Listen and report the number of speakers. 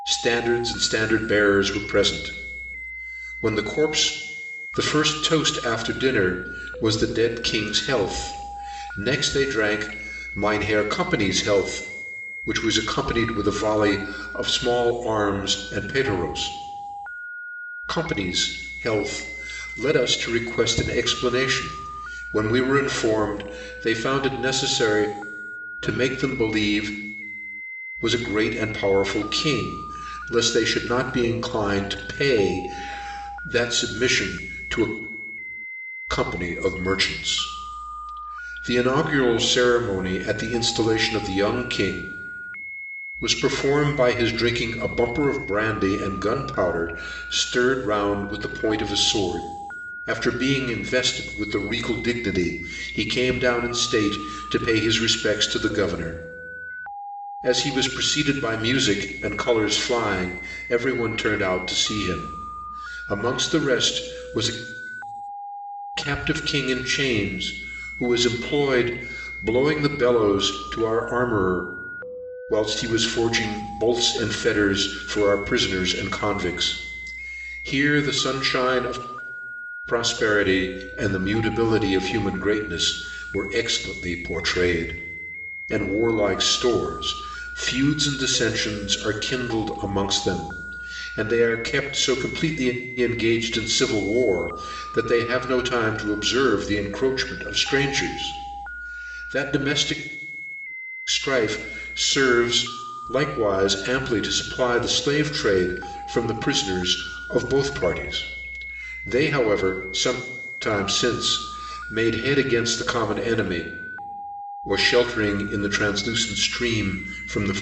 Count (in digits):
1